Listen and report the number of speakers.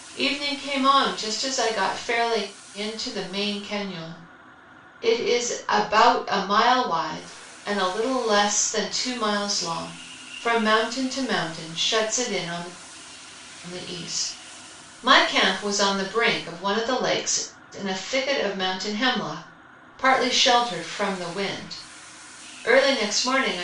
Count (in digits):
1